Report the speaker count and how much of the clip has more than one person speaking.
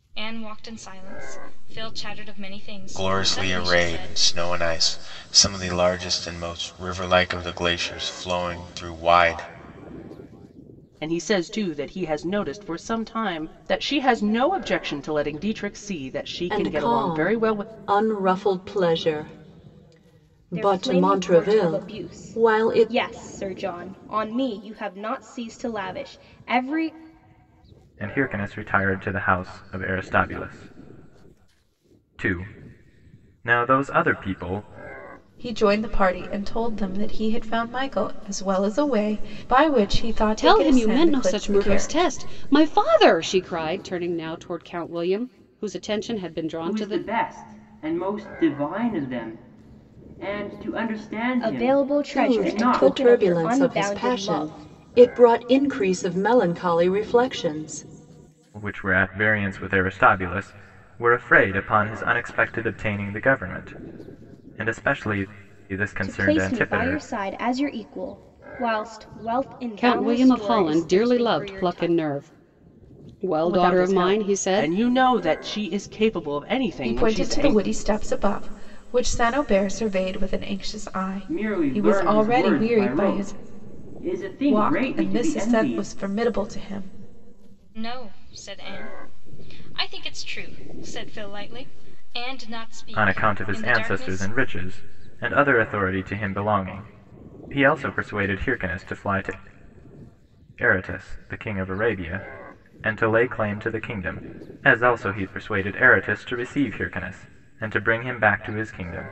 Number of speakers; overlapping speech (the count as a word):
nine, about 20%